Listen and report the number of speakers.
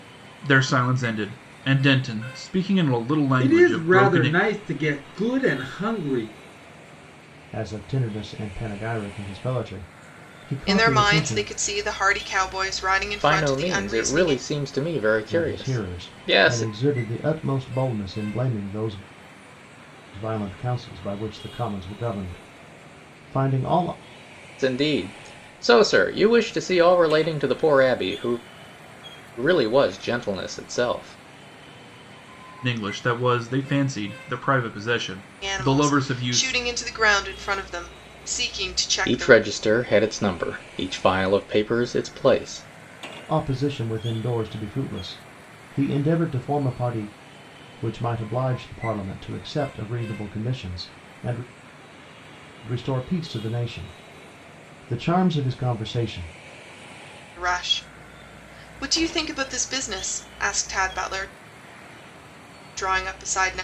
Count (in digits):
5